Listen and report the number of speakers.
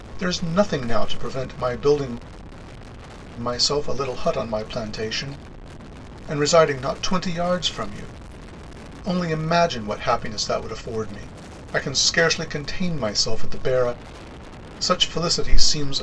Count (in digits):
1